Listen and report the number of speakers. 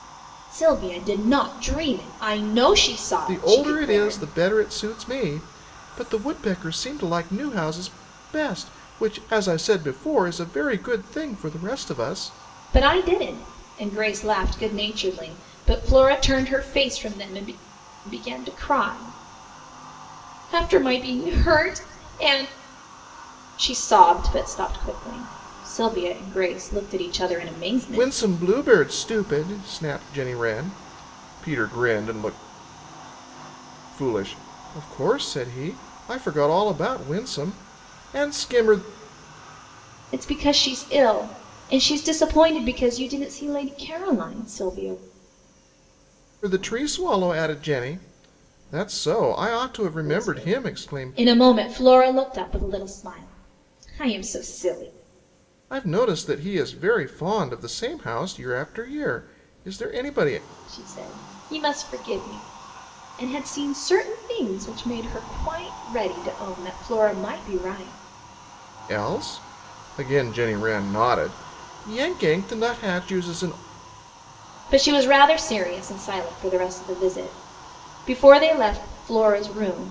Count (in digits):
2